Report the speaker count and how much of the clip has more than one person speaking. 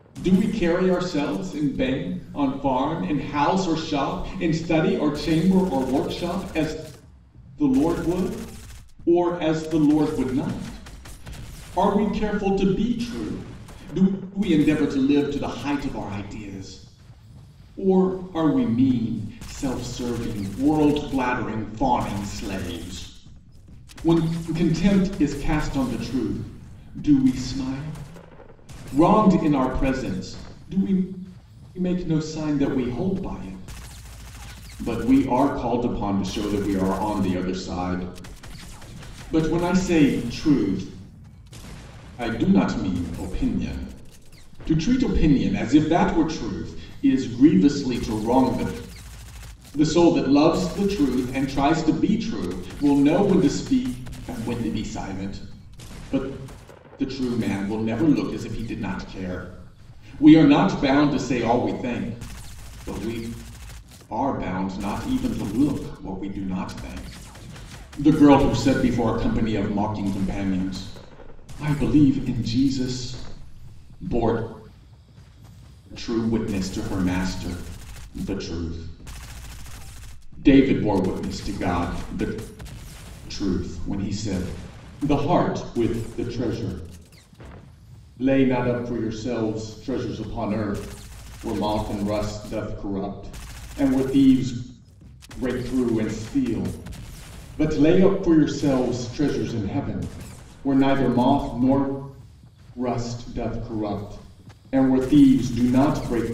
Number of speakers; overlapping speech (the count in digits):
1, no overlap